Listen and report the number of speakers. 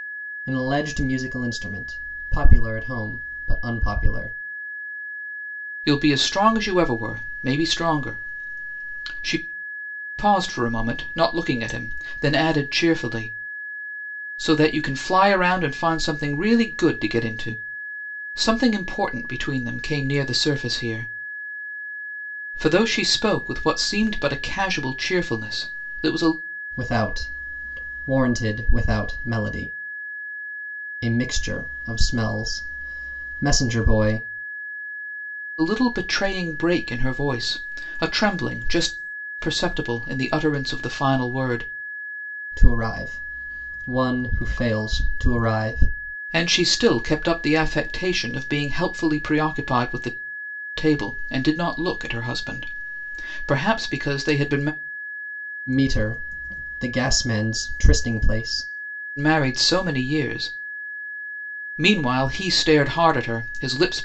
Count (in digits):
2